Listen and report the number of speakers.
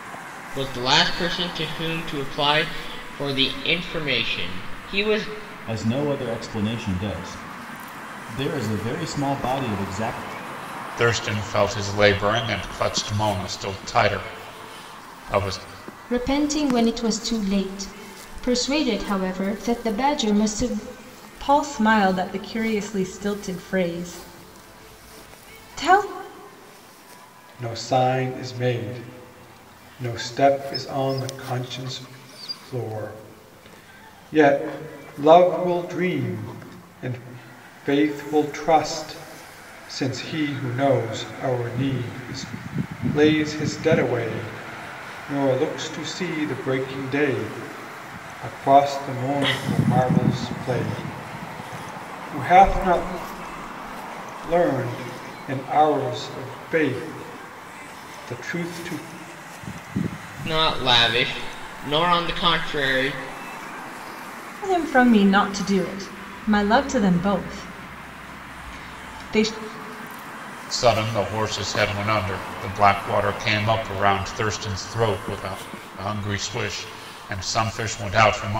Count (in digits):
6